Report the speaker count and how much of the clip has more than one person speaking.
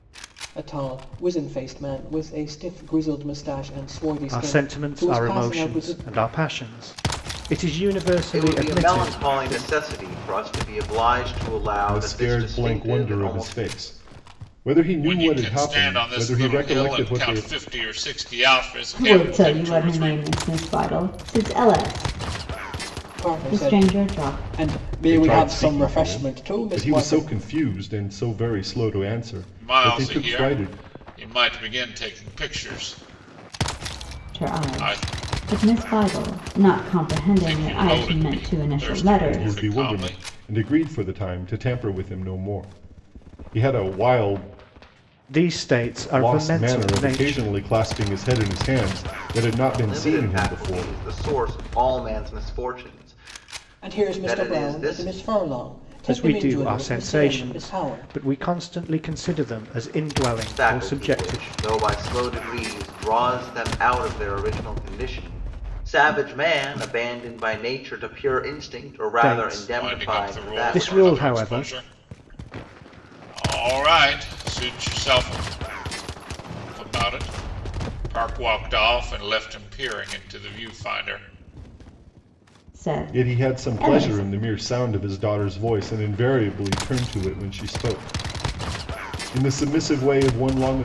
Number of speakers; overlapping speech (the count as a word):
six, about 31%